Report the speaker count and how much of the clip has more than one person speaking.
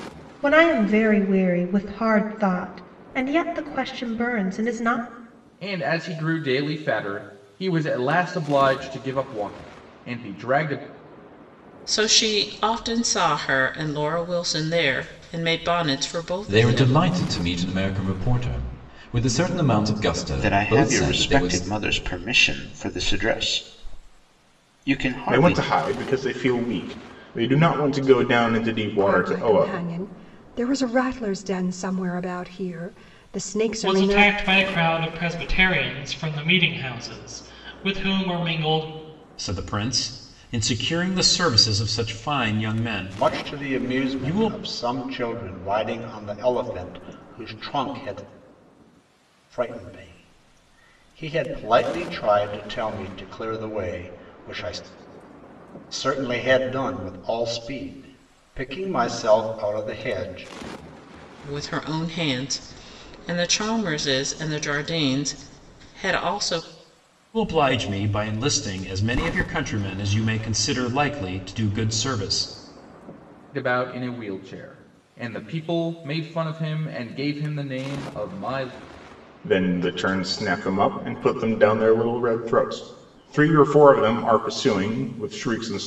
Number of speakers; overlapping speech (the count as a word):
ten, about 6%